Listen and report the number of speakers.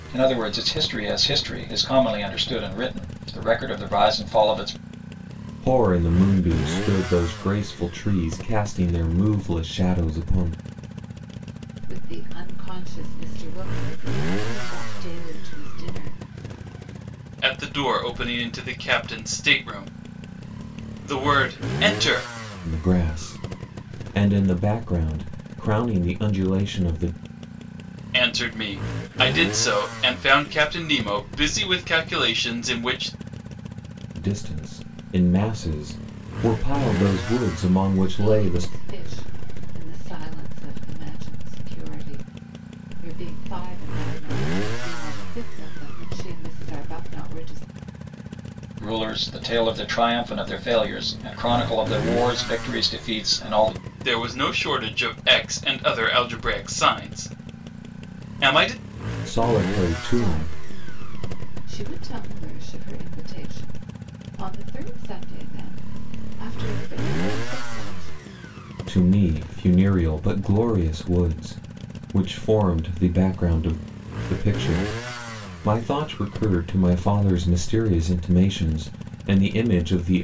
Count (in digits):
4